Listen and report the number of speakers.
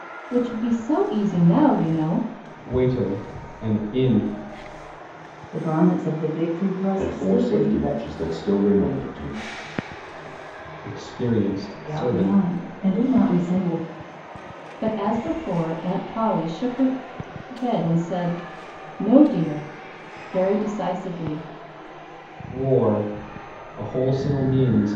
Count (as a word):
four